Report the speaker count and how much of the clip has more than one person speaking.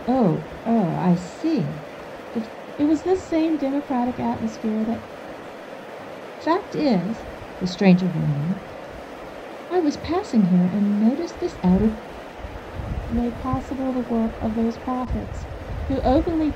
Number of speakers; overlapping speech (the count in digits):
2, no overlap